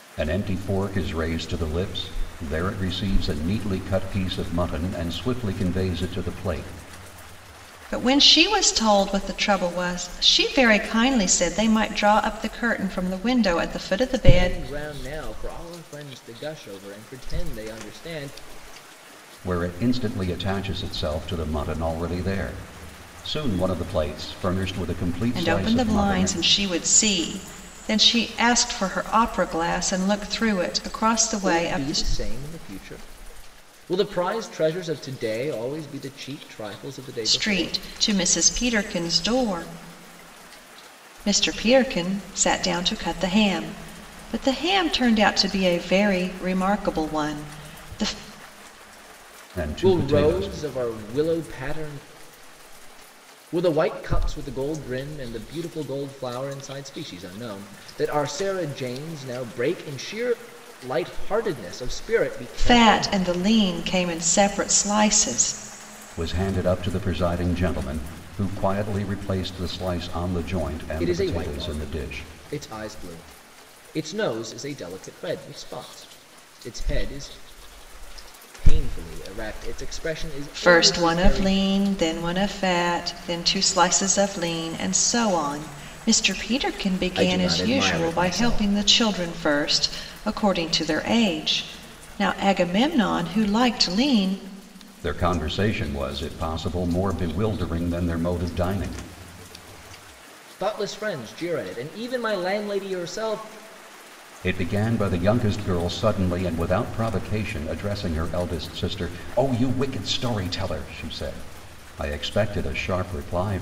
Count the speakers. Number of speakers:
3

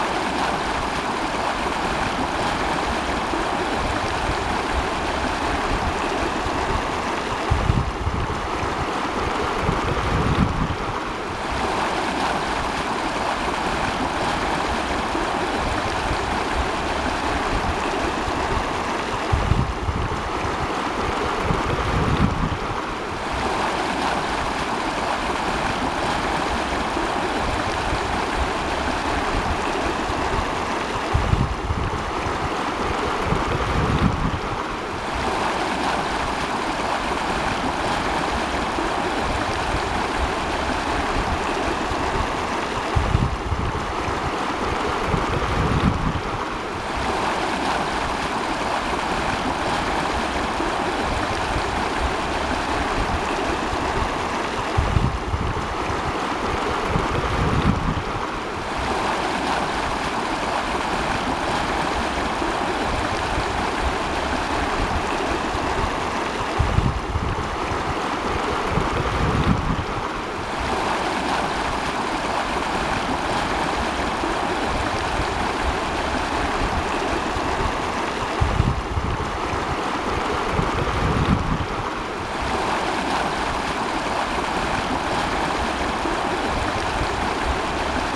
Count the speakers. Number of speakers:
0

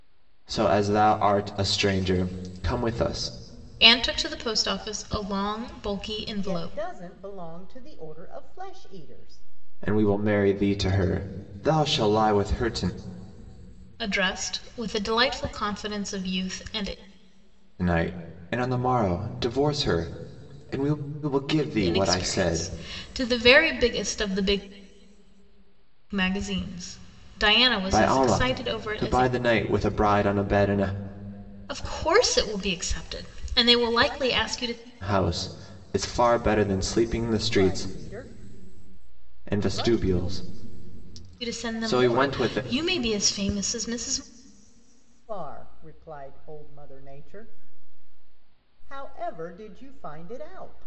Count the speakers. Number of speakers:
3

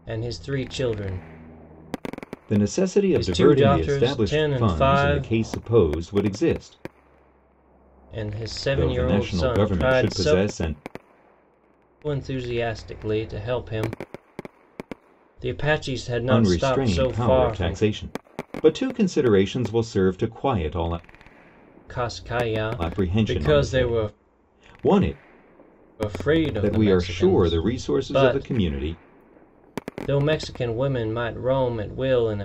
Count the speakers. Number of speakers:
2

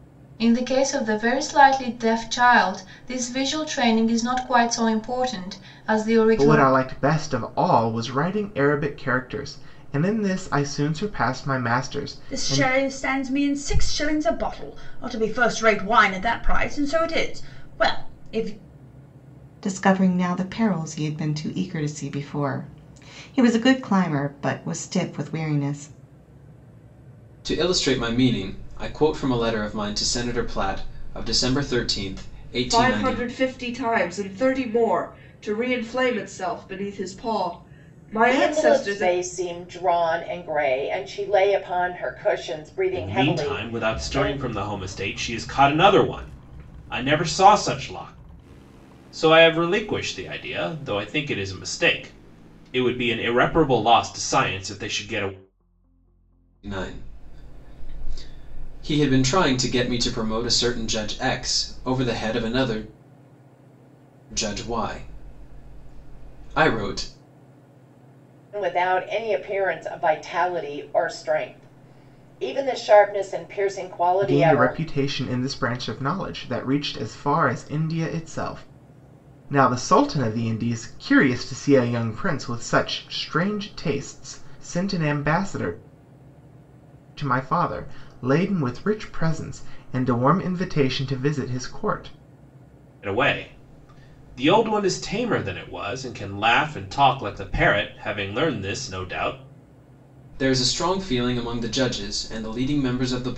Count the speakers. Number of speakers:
8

